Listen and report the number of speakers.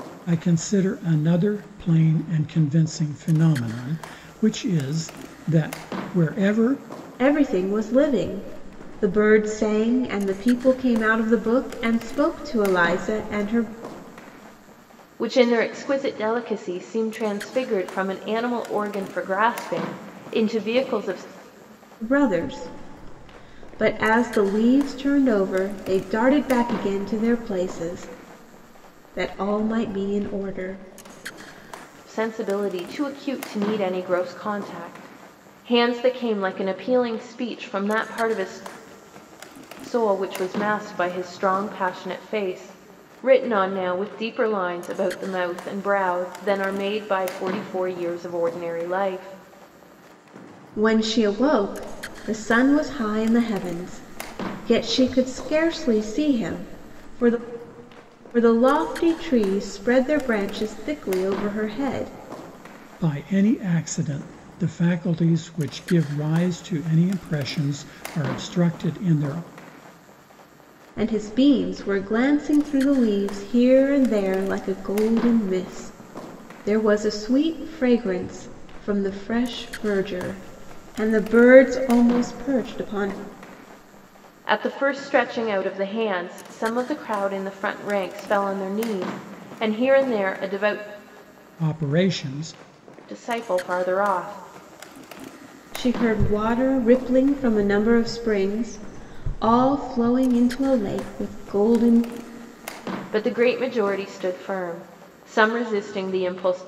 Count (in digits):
3